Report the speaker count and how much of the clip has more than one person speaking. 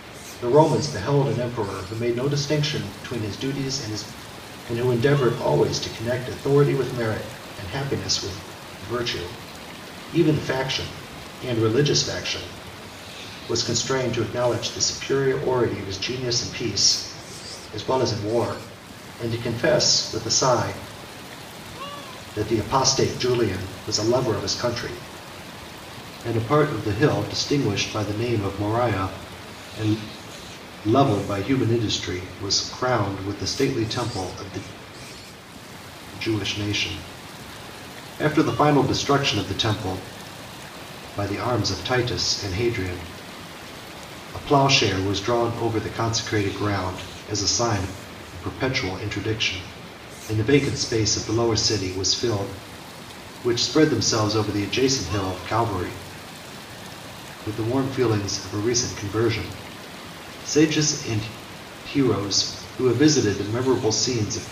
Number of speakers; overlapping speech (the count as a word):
one, no overlap